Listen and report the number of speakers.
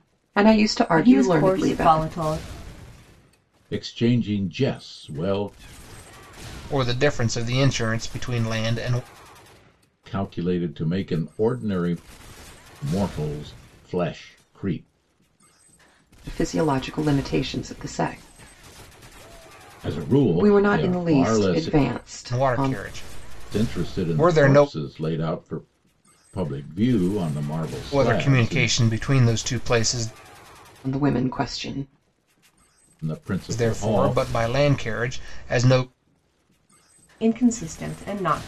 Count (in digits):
4